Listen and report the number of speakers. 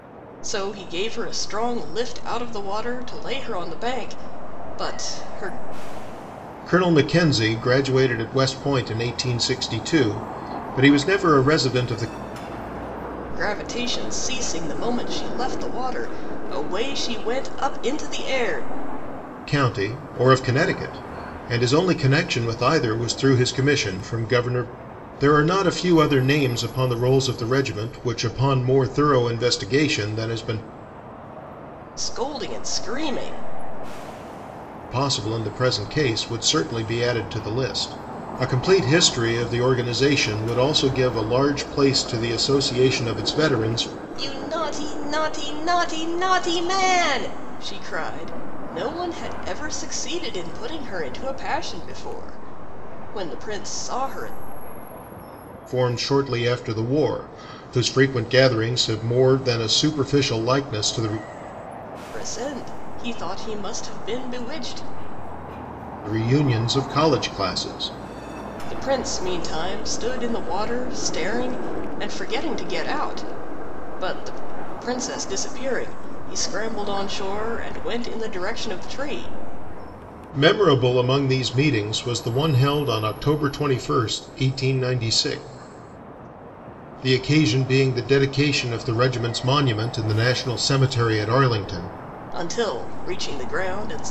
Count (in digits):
2